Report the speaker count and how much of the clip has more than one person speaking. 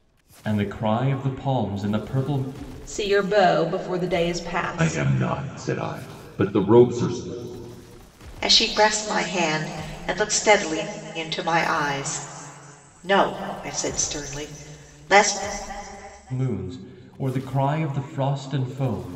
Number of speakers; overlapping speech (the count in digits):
4, about 2%